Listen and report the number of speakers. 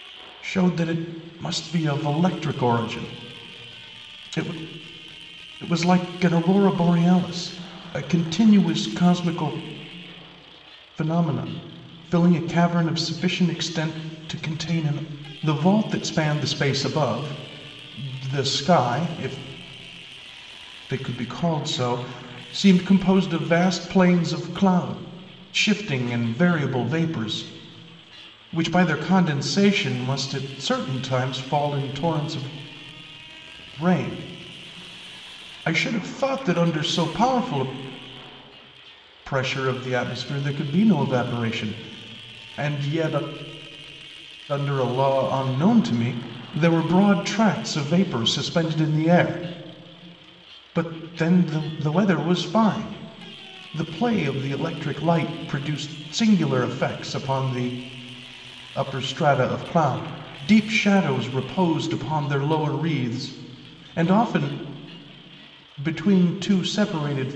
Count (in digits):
1